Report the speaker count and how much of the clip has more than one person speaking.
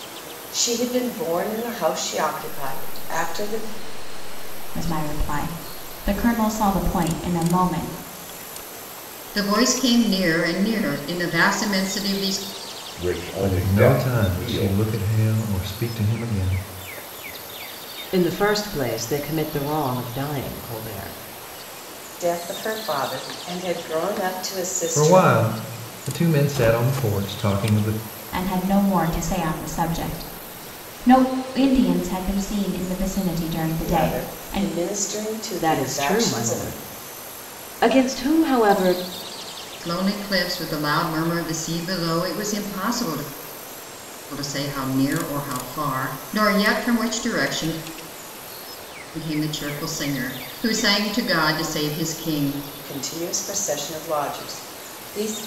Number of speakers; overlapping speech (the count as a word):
seven, about 11%